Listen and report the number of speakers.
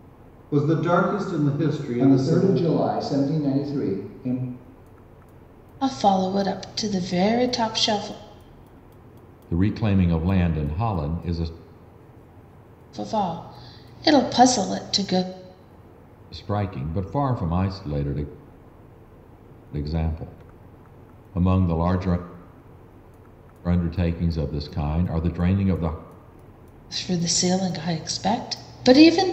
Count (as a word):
four